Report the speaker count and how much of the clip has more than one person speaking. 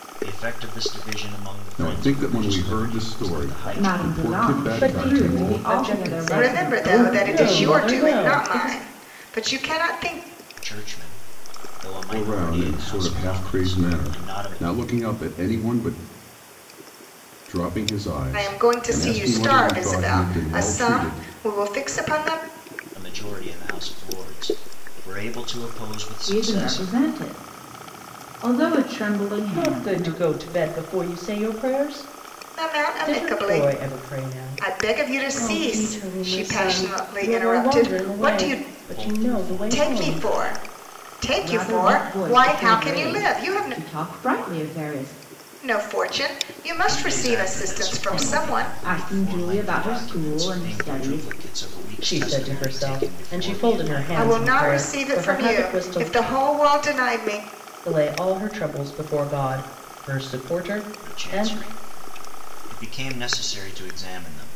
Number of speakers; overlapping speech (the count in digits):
5, about 50%